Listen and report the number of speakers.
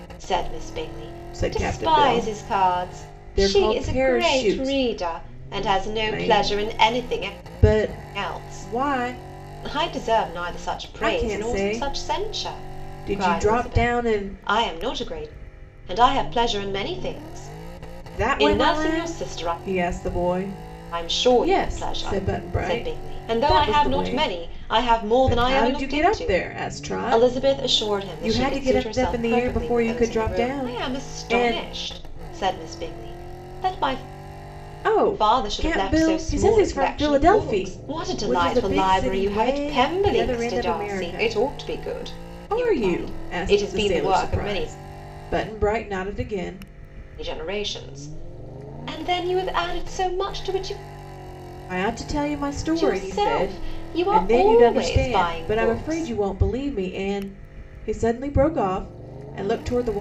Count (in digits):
2